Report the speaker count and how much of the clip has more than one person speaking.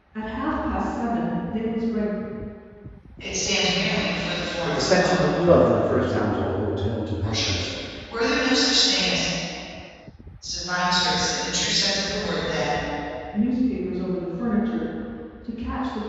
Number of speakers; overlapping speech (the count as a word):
four, about 16%